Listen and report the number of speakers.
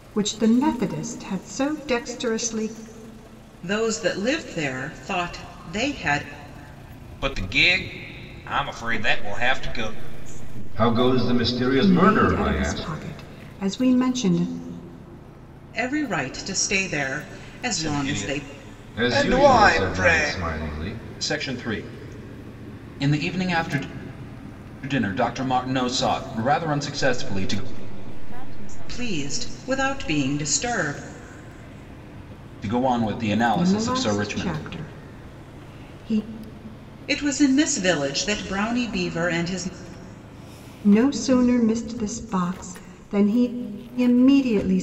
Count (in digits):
5